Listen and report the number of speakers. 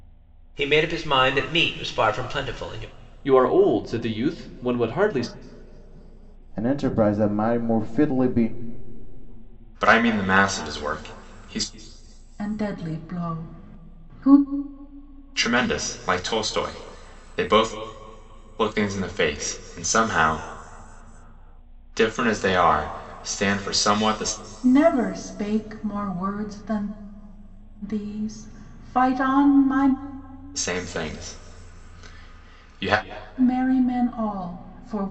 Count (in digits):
5